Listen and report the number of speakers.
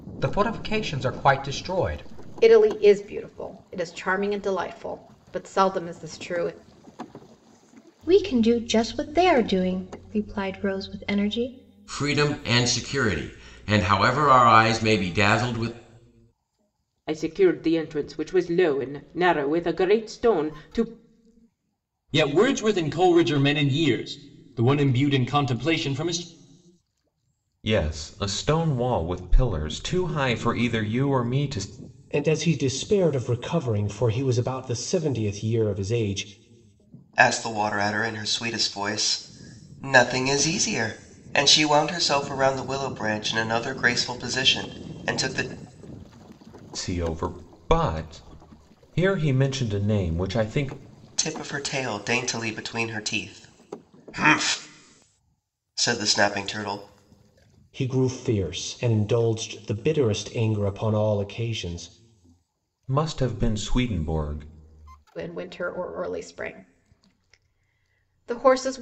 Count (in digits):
9